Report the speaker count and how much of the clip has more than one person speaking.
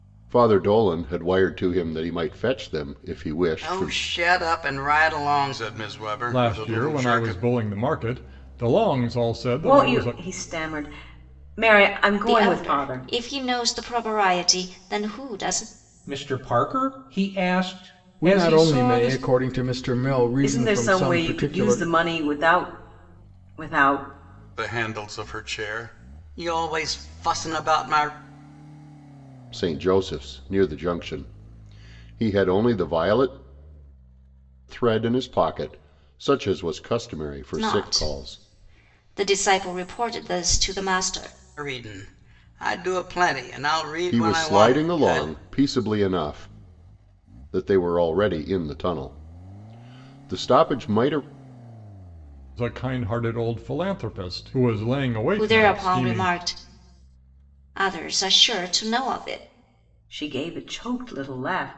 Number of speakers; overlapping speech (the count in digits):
7, about 14%